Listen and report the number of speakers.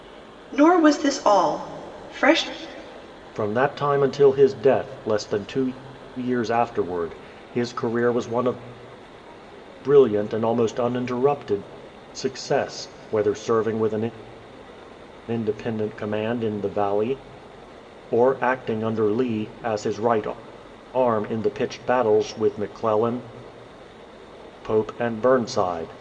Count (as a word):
two